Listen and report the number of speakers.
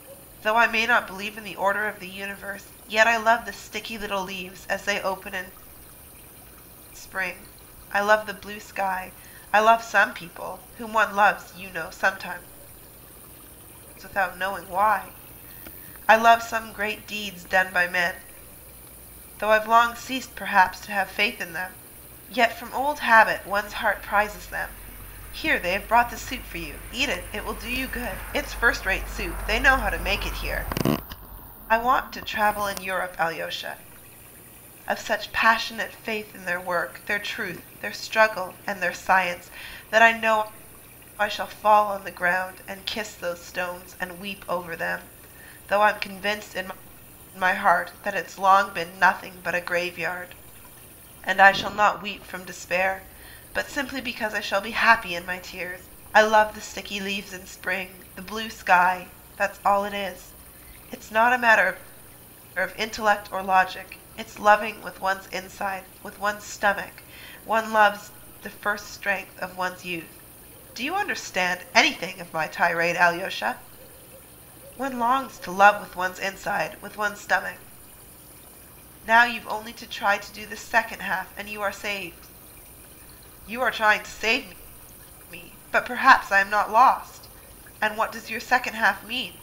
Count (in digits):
1